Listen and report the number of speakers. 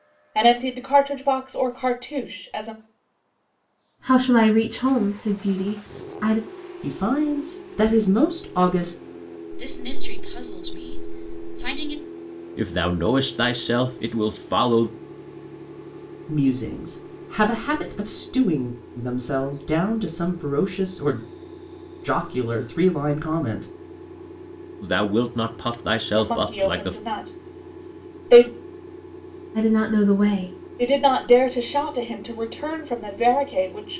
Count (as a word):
five